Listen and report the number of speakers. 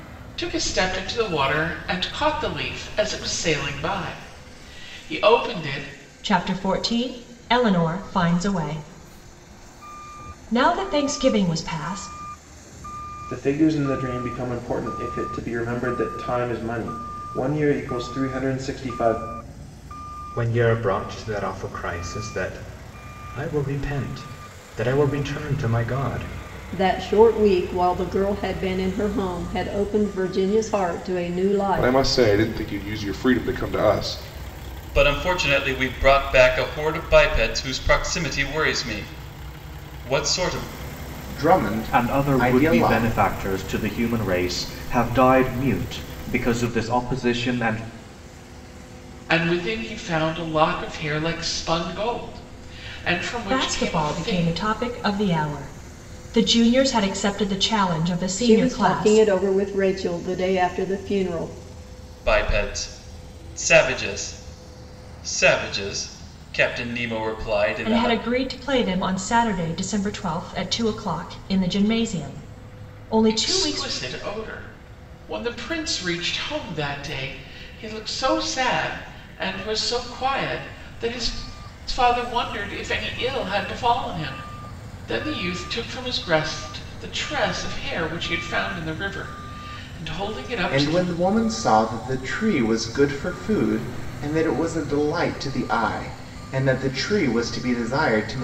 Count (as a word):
nine